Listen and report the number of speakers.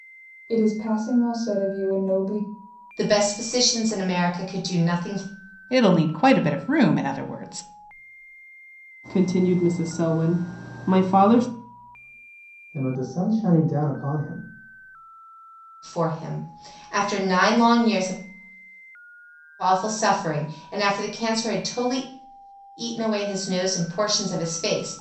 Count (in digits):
5